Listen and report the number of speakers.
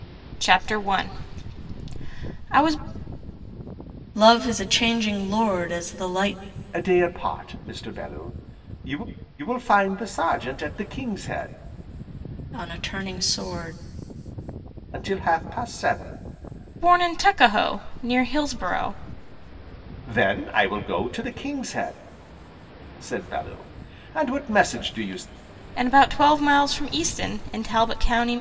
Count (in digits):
3